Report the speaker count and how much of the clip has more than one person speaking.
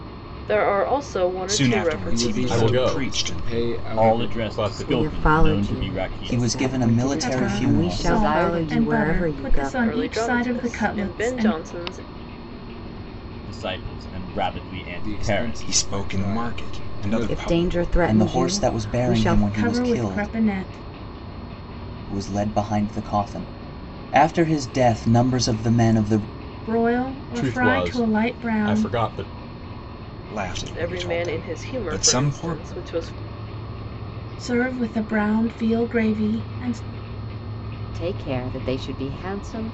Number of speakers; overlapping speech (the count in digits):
9, about 47%